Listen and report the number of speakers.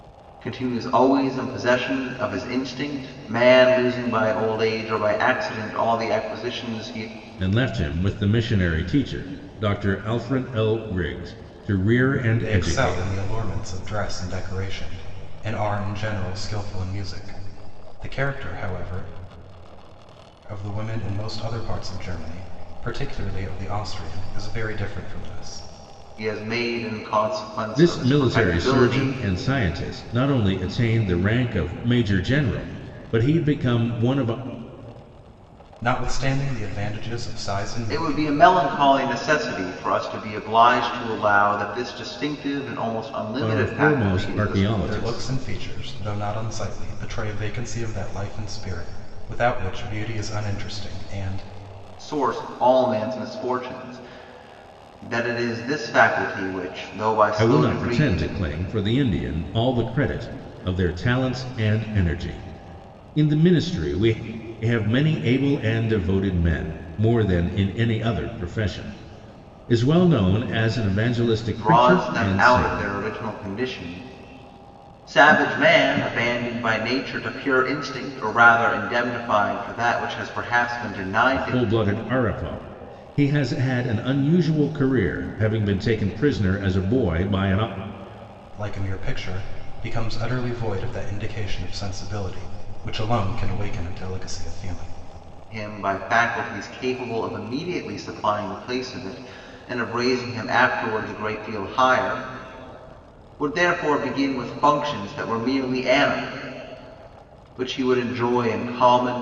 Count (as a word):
three